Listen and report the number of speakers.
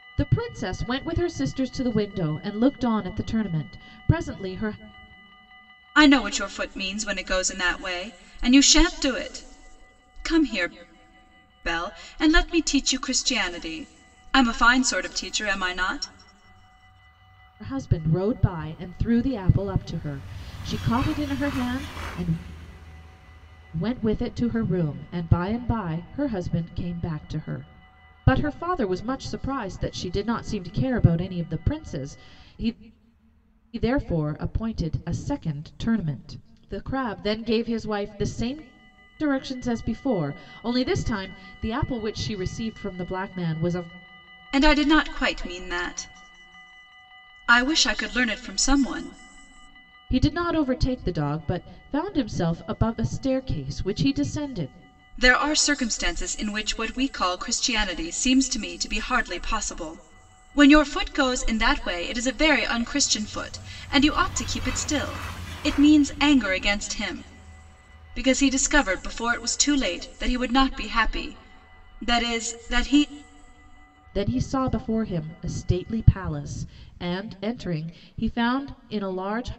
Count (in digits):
2